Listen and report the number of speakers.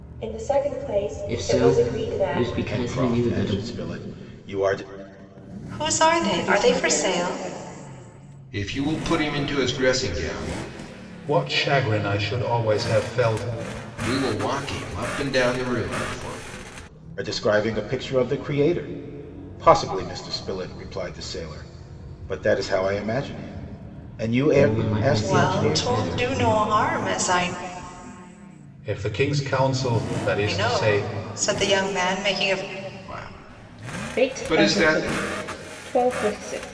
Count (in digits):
7